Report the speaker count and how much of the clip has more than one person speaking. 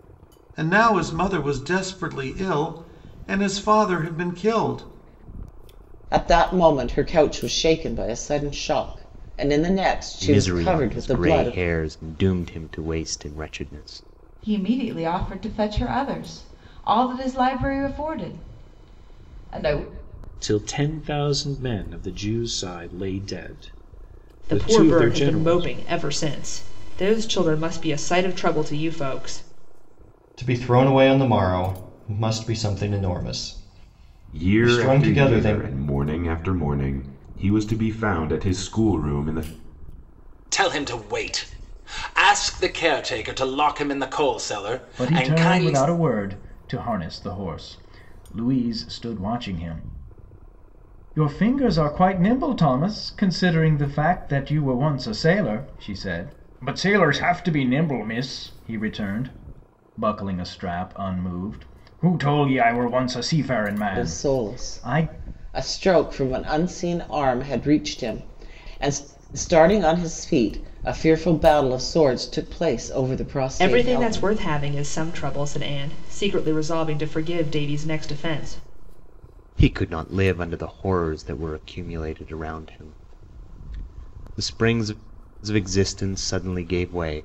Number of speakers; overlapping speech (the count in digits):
10, about 8%